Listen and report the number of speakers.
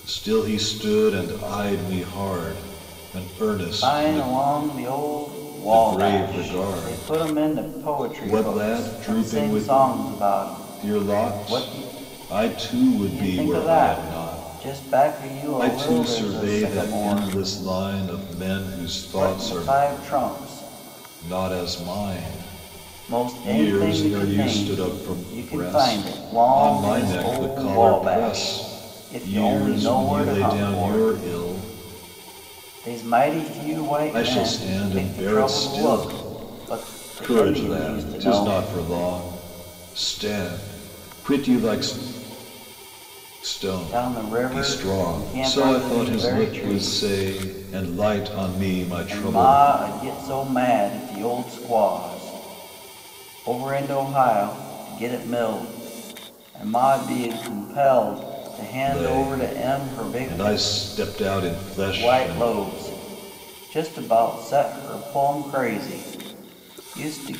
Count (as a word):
two